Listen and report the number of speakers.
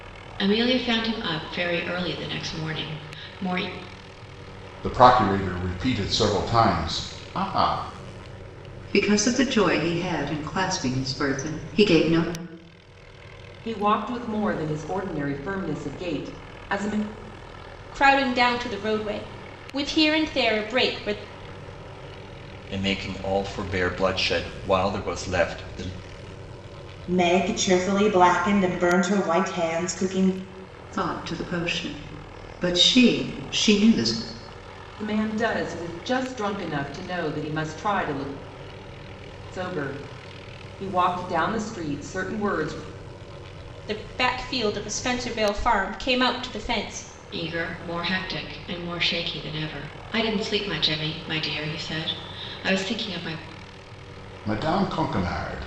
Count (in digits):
7